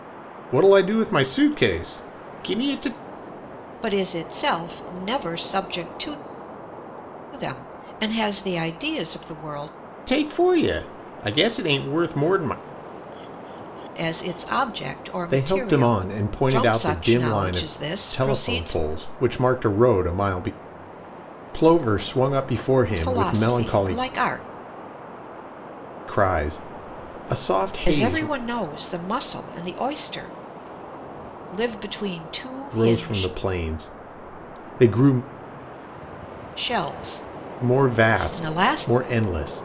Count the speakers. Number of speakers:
2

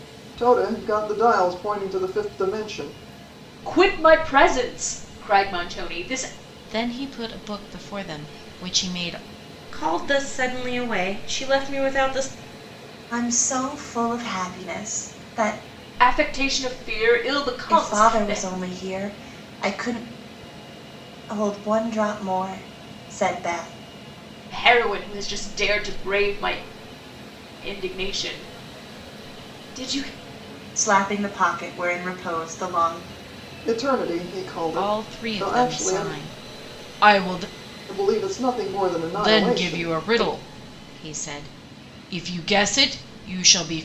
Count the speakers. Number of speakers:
5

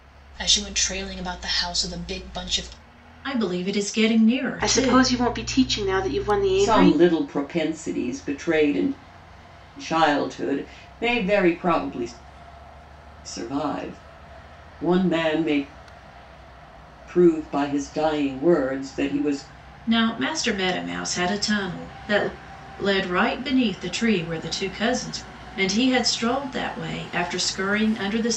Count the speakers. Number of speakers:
4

